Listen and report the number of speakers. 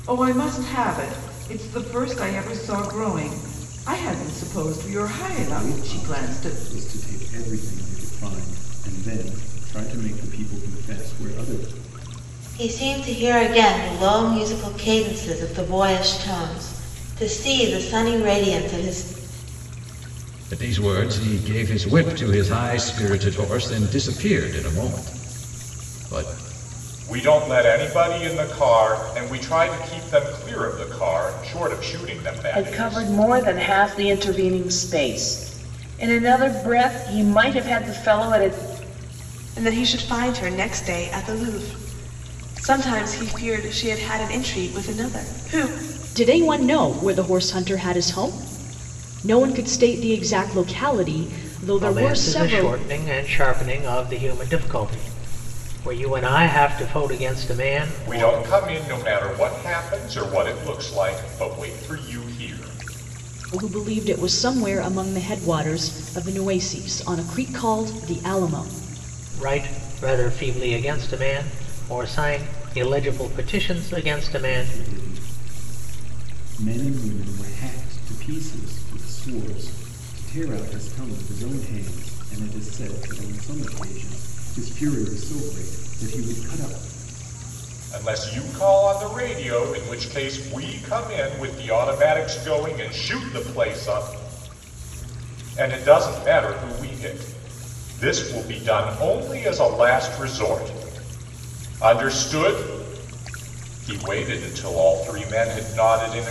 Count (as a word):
nine